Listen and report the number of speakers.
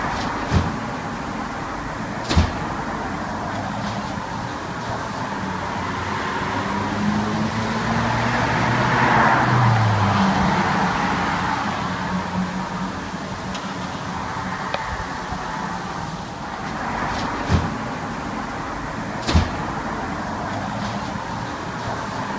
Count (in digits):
0